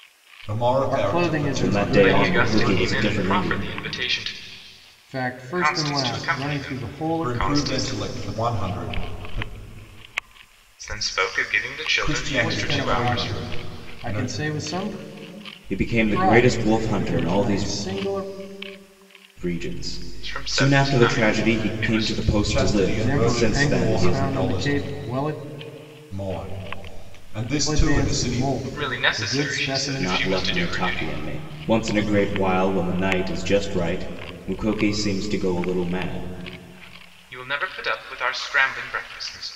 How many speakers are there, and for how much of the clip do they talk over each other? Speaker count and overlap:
4, about 43%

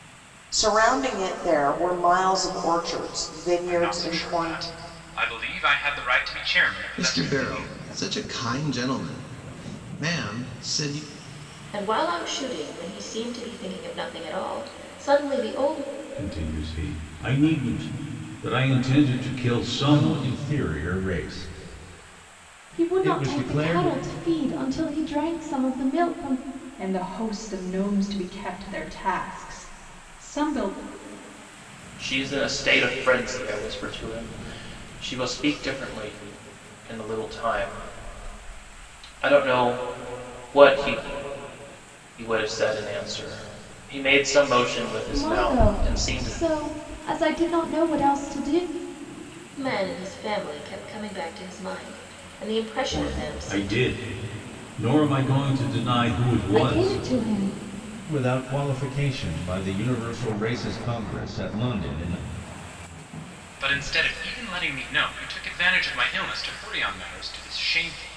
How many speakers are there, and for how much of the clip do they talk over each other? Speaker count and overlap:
9, about 9%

